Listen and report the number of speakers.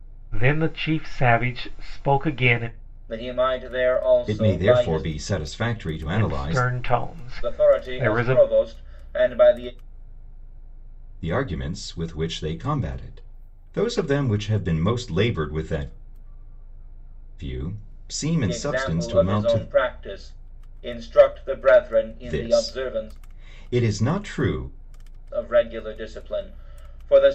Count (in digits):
3